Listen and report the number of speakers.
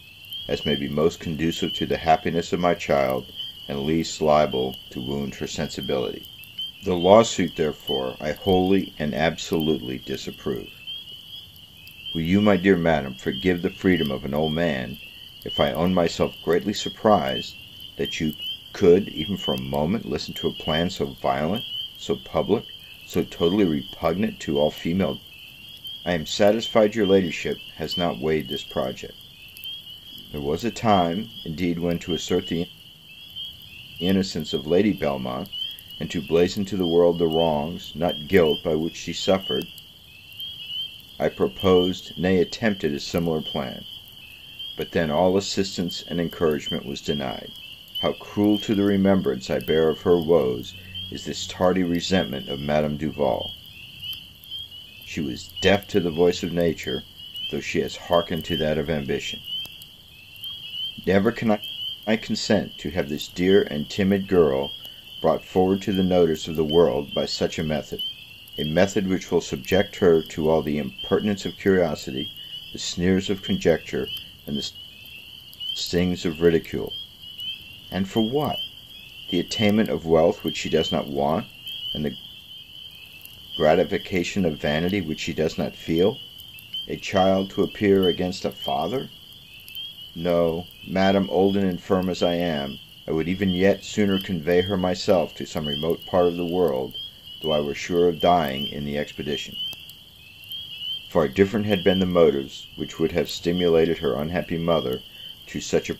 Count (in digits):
1